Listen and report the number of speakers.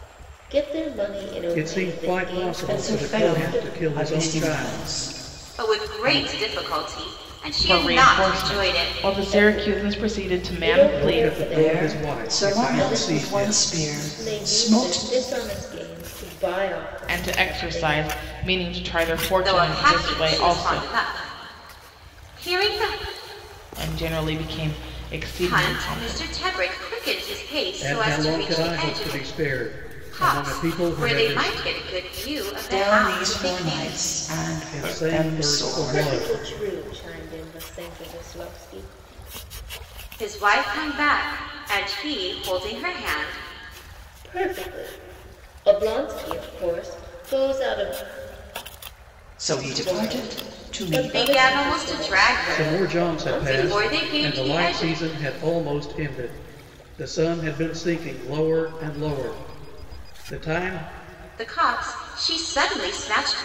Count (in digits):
5